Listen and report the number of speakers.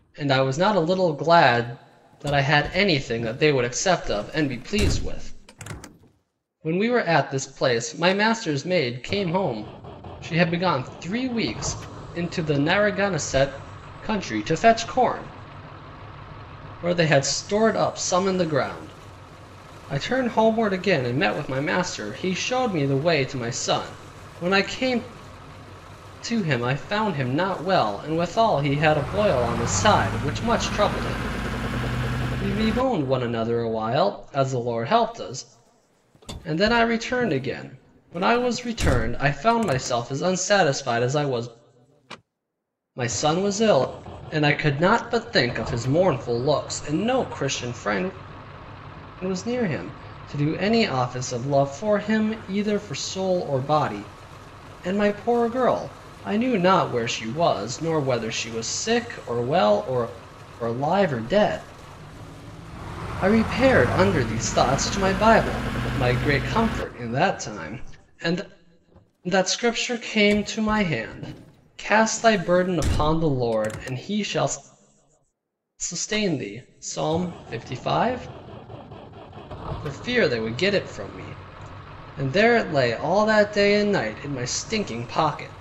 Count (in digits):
1